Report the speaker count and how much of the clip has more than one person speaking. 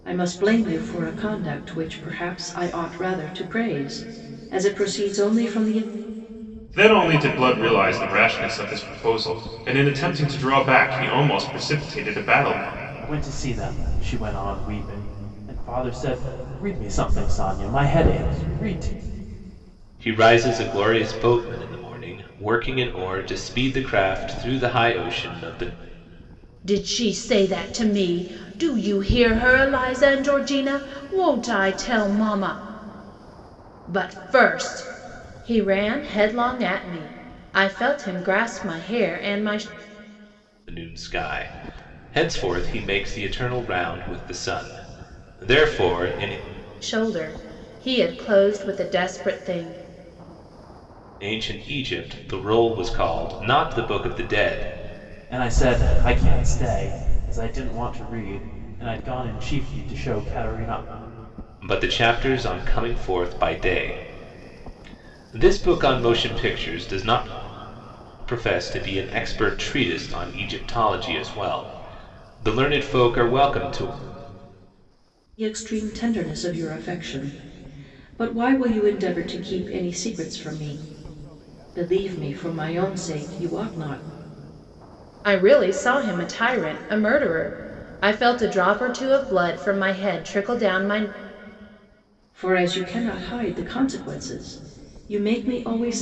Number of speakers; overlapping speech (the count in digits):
5, no overlap